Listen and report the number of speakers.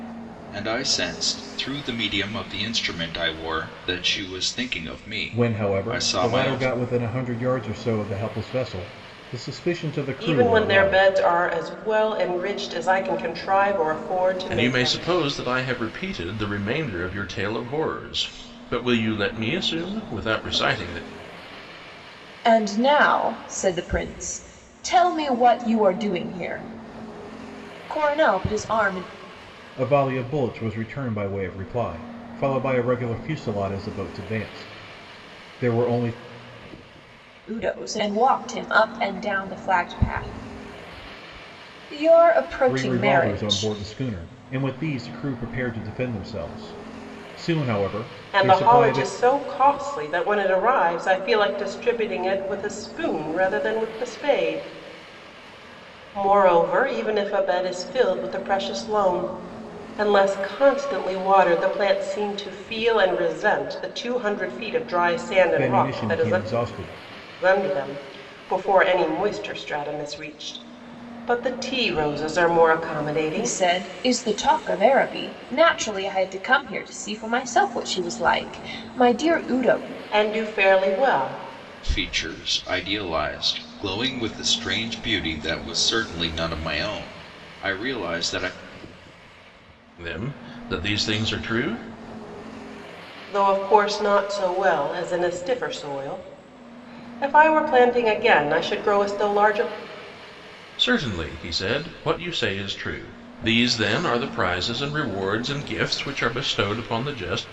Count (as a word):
five